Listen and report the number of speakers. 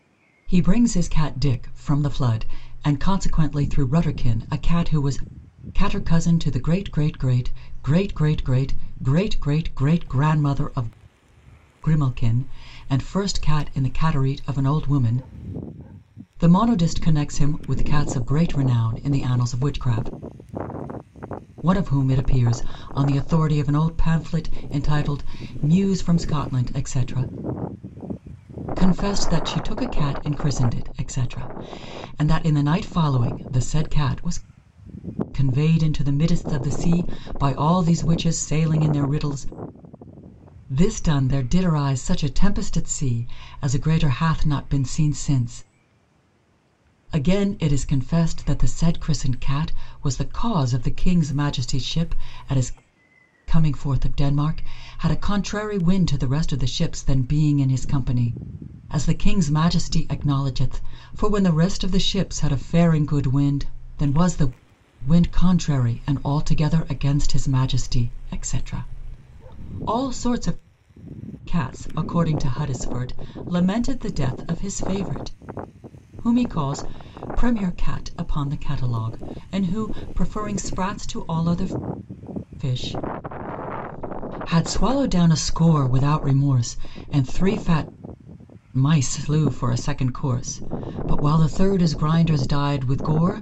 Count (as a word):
one